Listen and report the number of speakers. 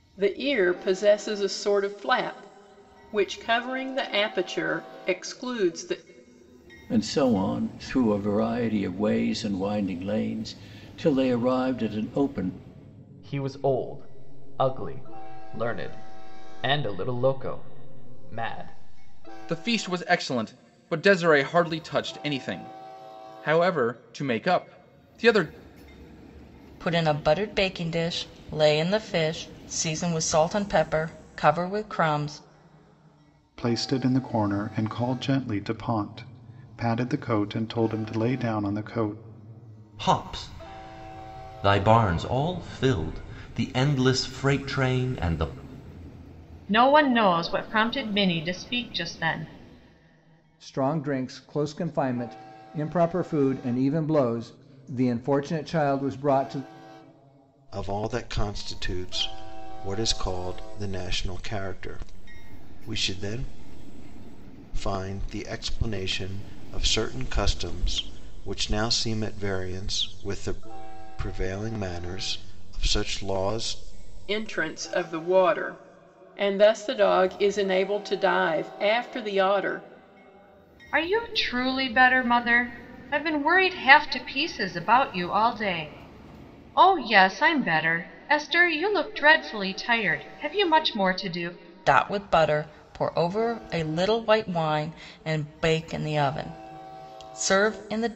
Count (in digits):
10